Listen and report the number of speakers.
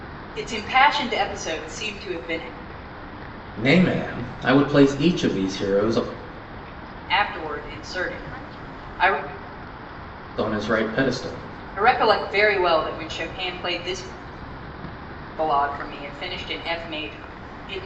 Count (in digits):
2